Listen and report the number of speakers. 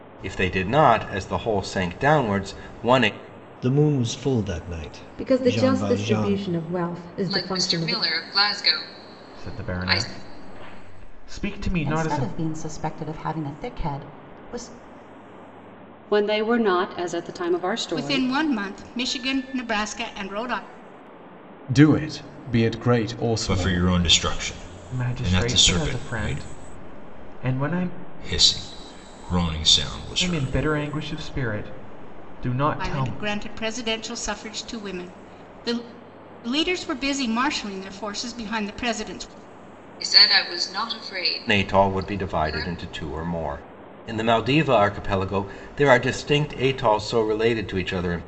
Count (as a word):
ten